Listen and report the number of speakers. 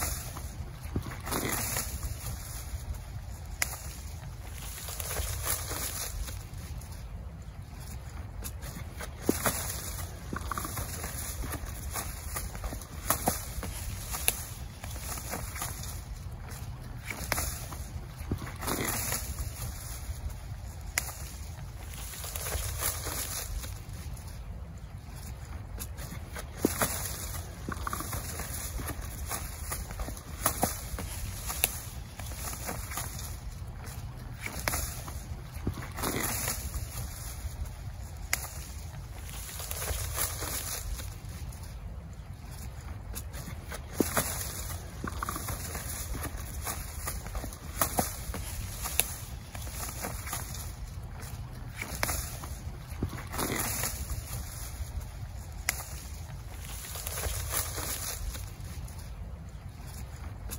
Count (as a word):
zero